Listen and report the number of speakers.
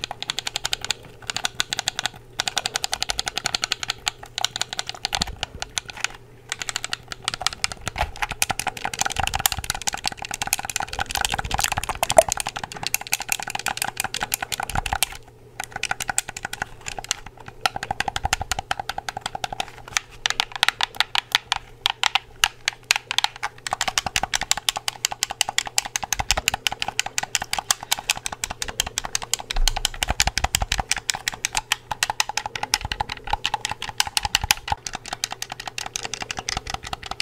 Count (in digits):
0